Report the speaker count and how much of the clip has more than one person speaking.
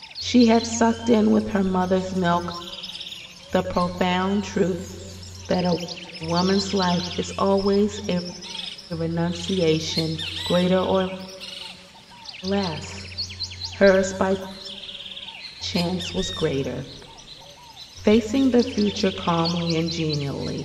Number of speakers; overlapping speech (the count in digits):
1, no overlap